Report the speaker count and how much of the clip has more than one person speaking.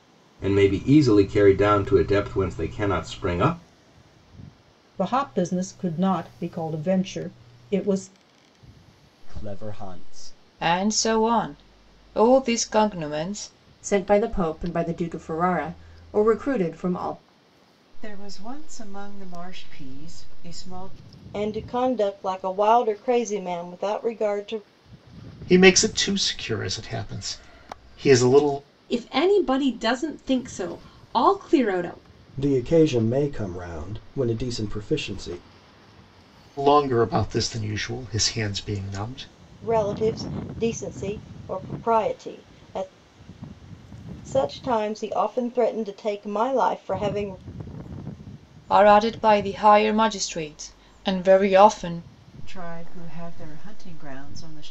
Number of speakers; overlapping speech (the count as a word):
ten, no overlap